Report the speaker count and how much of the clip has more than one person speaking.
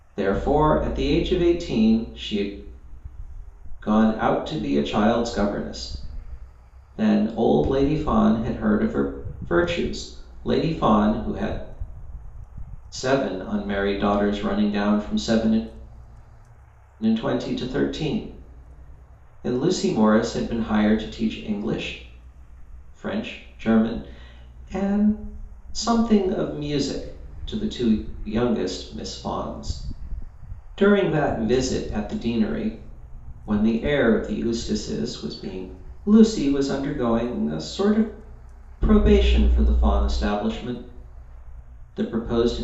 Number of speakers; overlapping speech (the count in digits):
1, no overlap